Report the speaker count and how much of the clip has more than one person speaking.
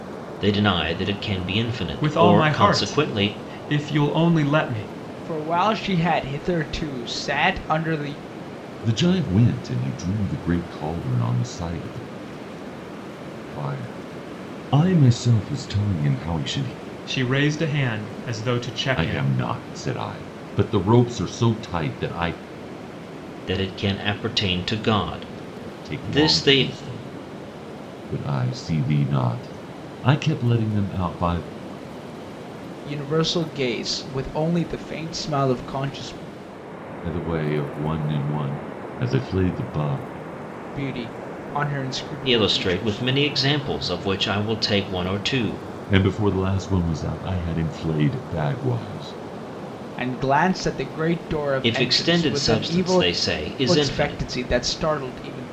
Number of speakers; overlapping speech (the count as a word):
four, about 10%